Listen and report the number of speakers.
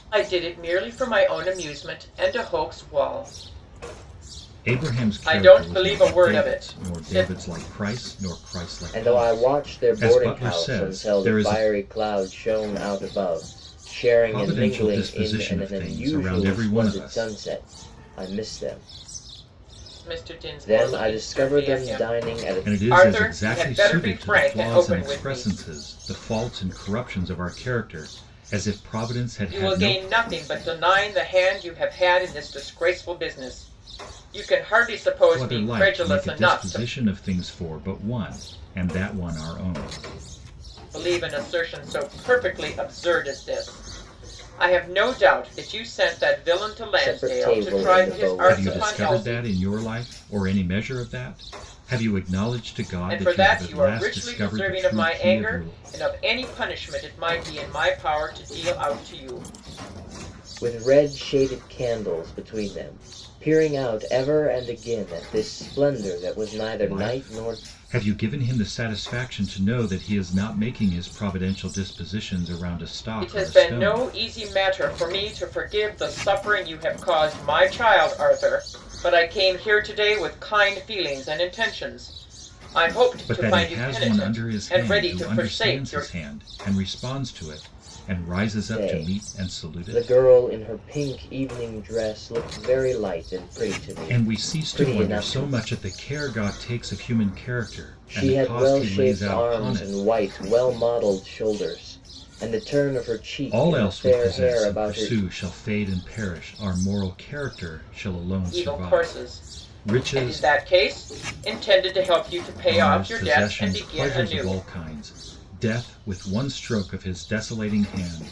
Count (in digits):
3